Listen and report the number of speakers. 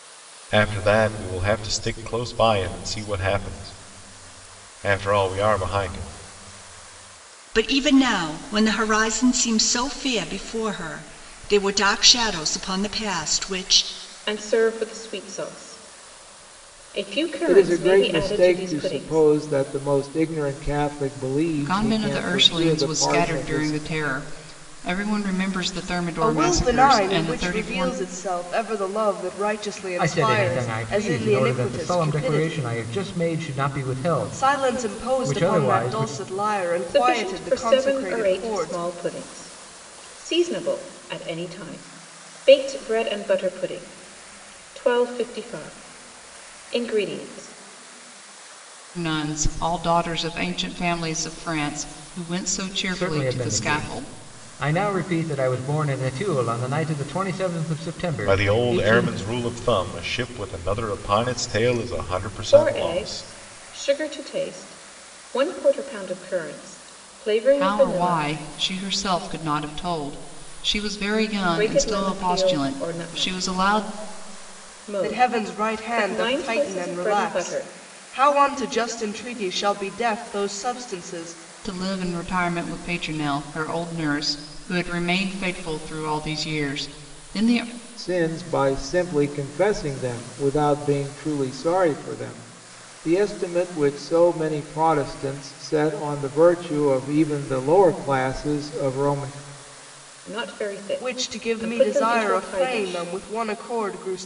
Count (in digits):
7